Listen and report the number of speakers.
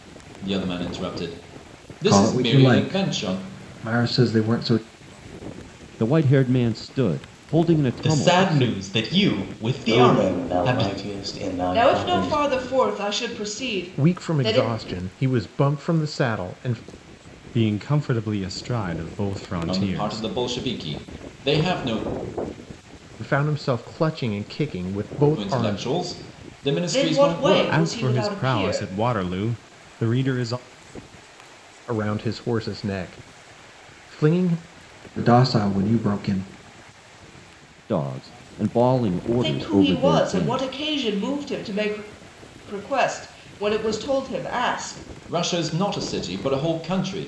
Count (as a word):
eight